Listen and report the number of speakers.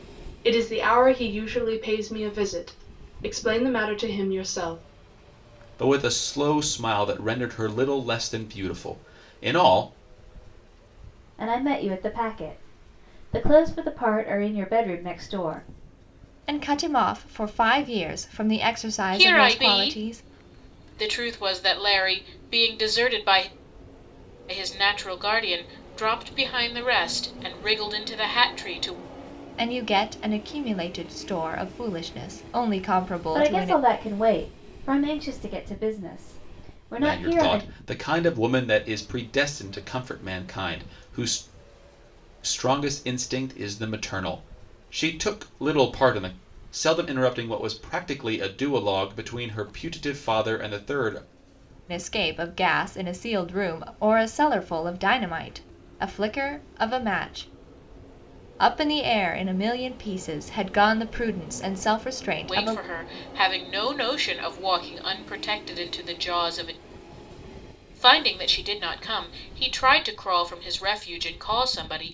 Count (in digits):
5